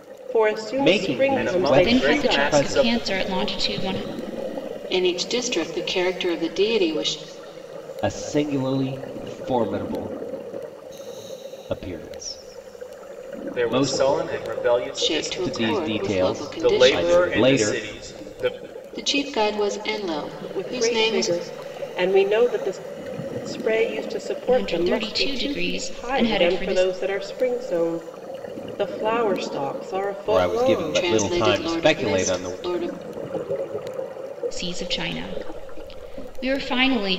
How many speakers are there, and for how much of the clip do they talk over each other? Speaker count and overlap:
five, about 32%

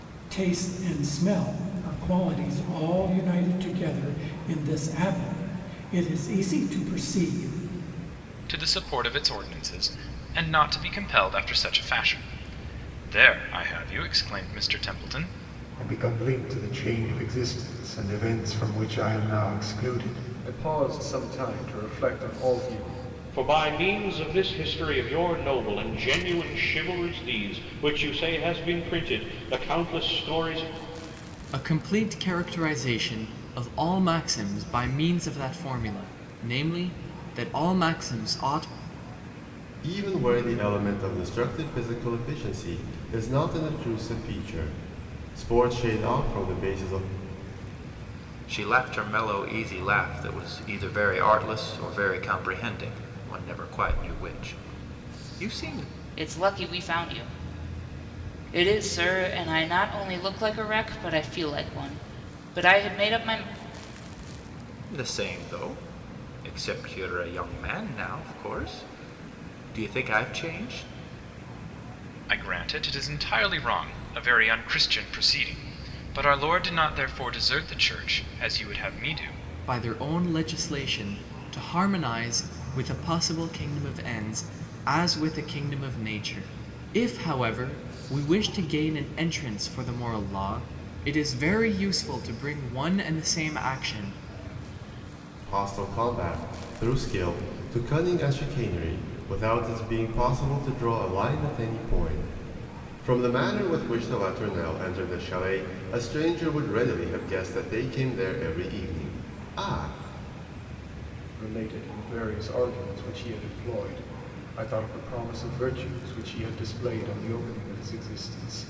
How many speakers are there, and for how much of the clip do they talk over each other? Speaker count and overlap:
eight, no overlap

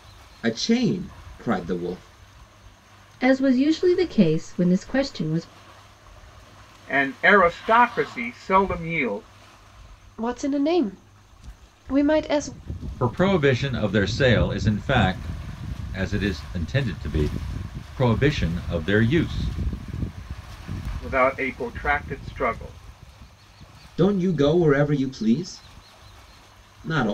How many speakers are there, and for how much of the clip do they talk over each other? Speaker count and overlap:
five, no overlap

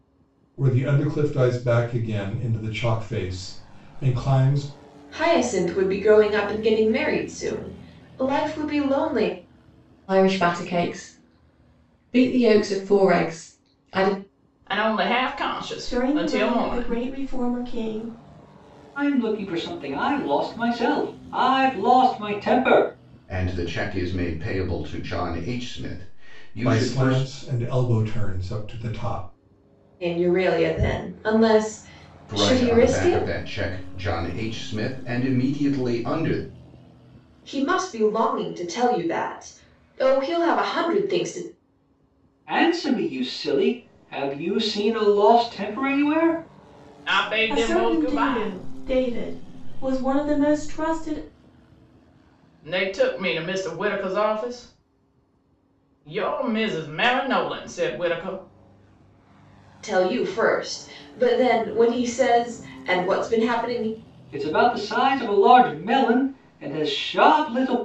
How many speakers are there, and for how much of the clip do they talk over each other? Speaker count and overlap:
seven, about 6%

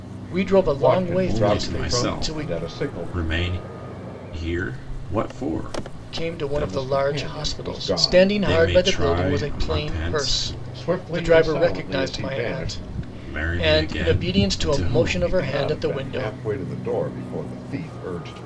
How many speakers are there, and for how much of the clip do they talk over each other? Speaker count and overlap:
three, about 66%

